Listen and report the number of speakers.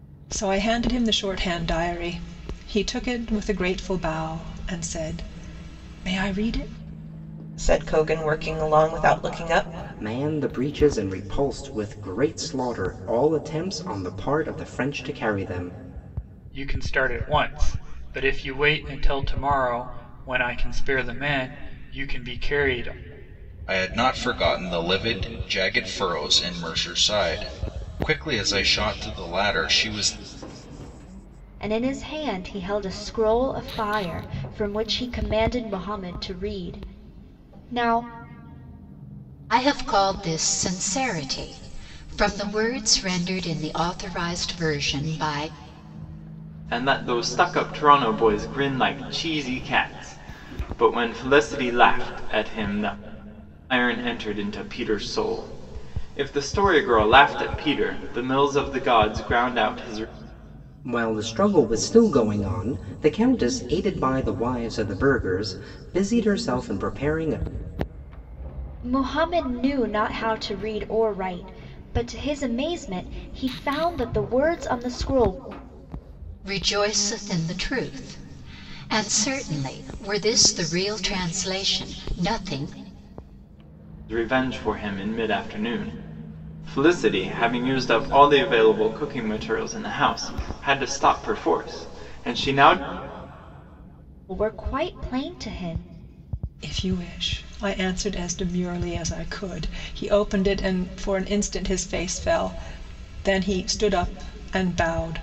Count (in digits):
8